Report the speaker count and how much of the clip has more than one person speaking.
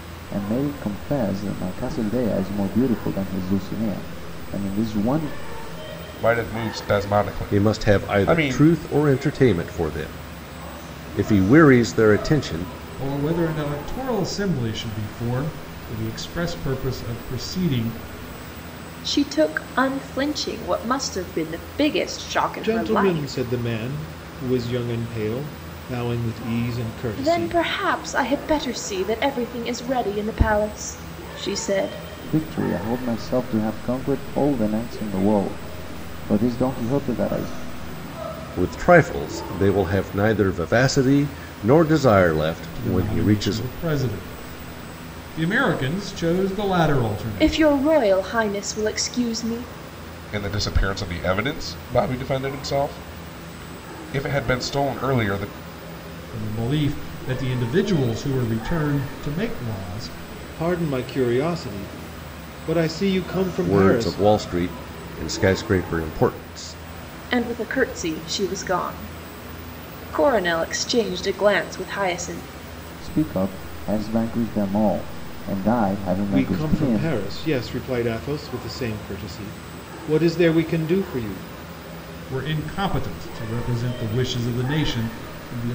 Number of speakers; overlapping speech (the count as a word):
six, about 6%